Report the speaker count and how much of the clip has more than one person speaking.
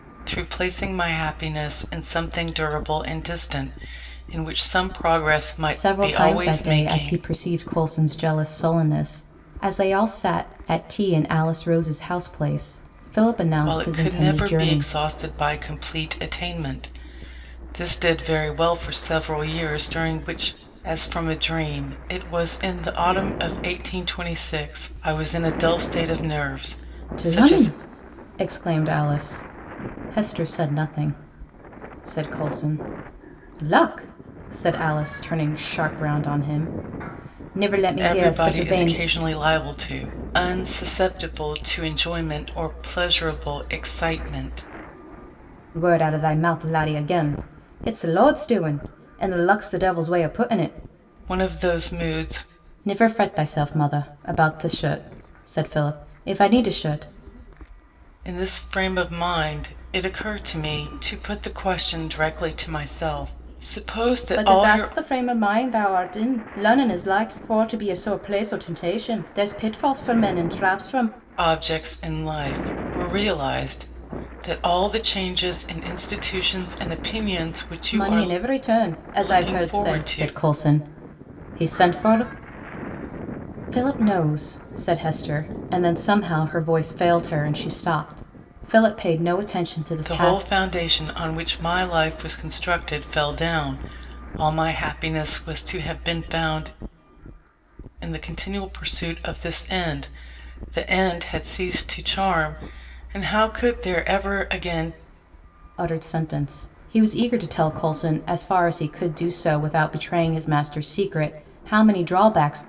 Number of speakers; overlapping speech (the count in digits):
2, about 6%